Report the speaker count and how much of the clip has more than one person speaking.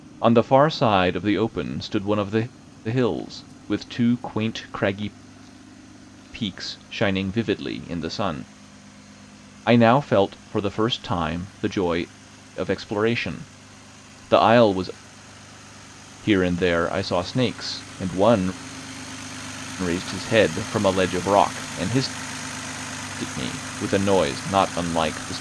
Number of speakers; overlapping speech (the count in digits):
1, no overlap